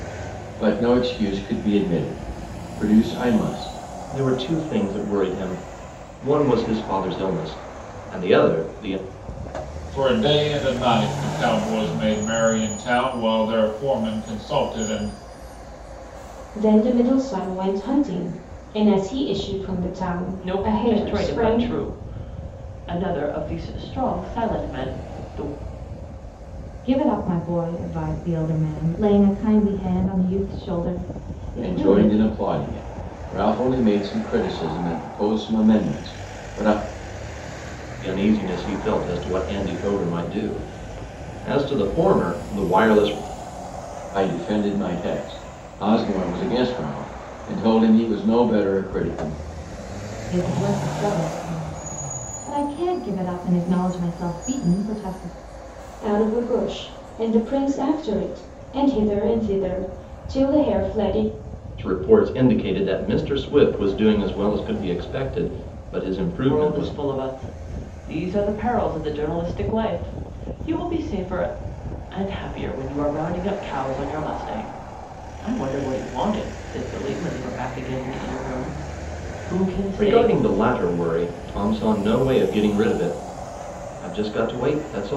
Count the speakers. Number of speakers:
6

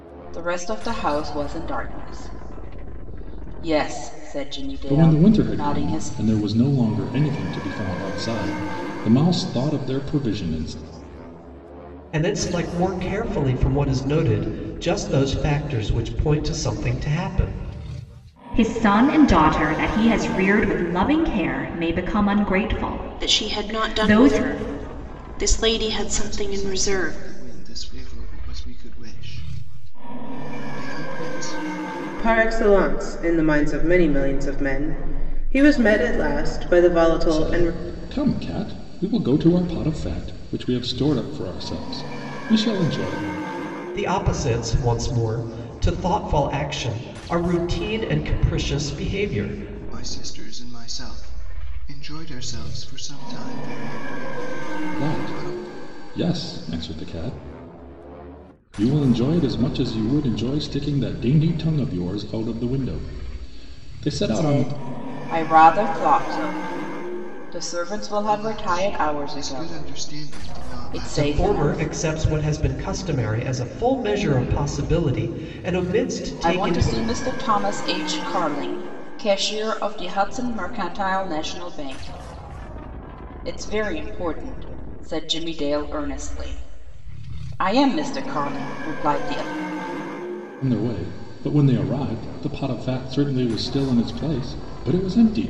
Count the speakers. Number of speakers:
7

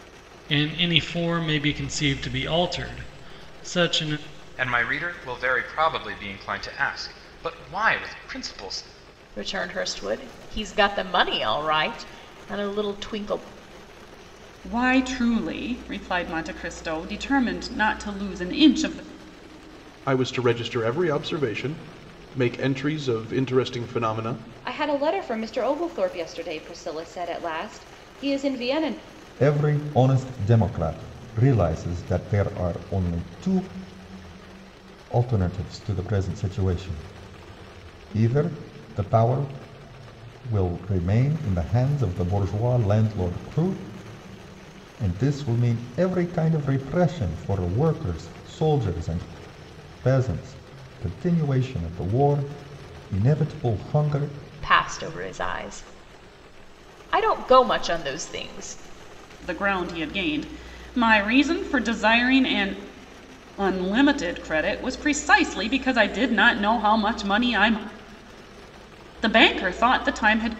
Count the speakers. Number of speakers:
7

